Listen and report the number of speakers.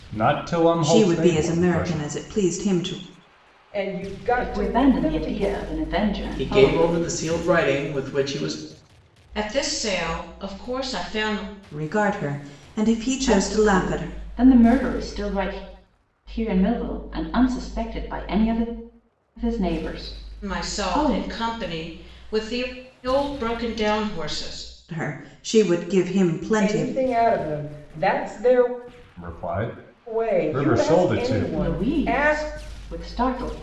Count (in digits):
6